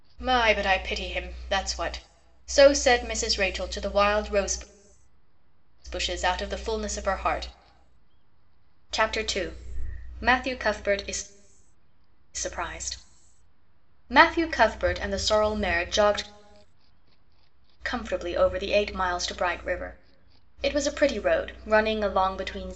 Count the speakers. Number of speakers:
one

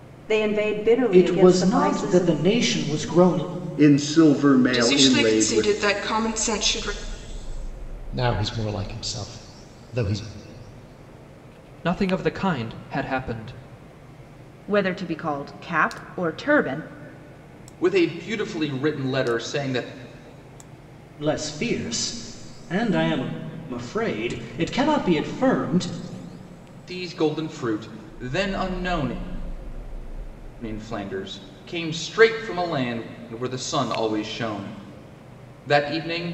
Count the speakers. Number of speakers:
eight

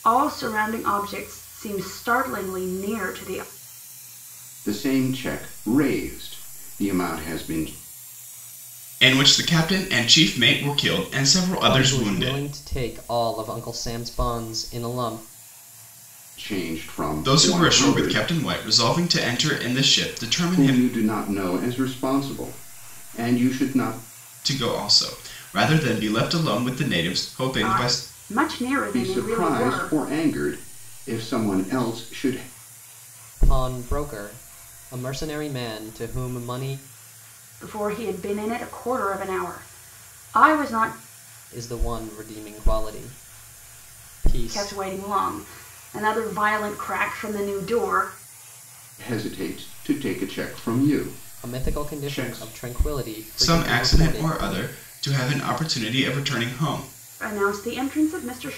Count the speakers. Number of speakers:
four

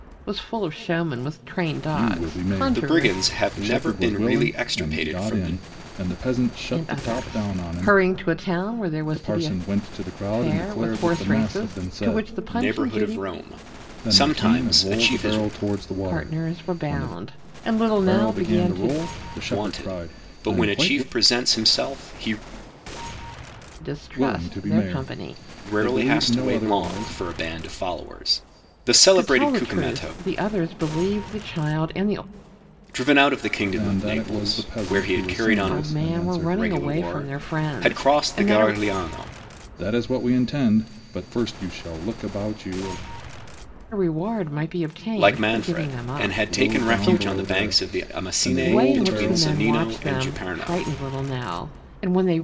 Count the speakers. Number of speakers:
three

